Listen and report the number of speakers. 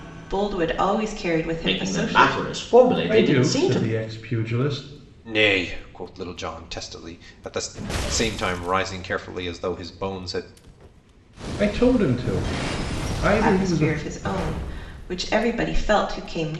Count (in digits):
4